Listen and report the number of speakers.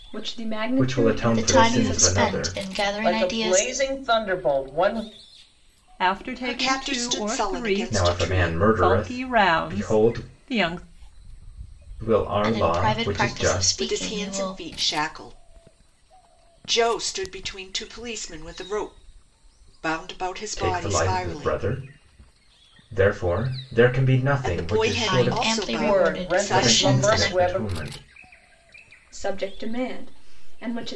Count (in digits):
6